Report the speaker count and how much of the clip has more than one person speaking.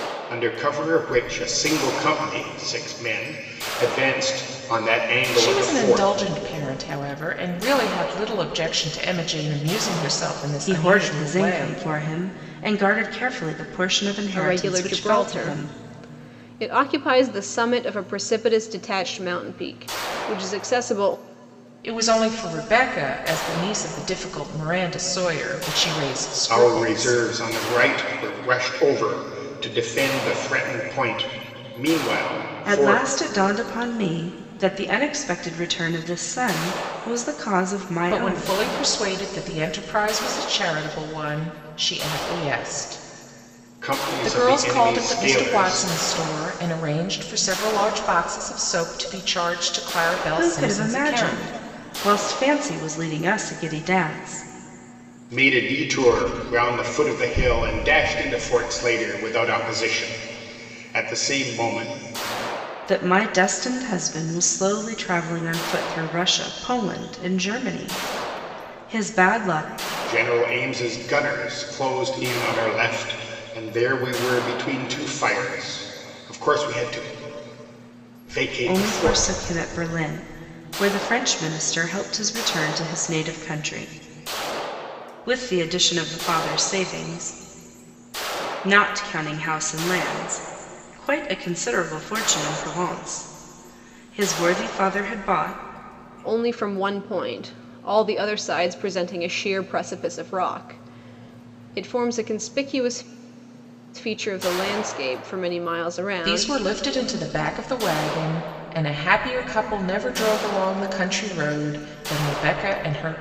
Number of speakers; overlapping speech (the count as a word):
four, about 8%